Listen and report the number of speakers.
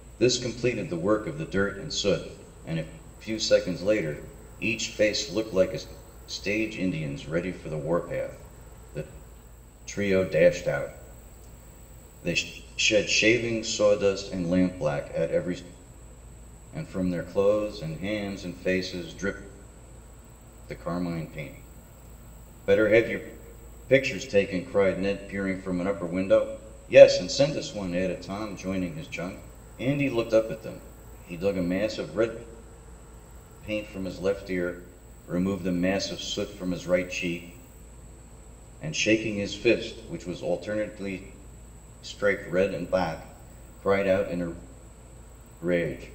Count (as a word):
one